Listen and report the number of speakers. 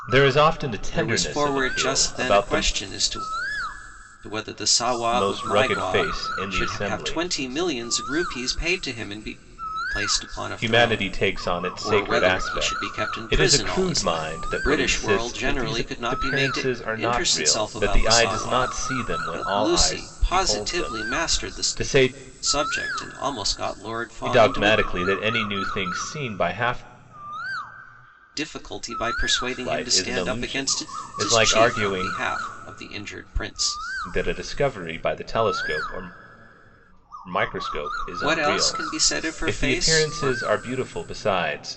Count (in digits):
2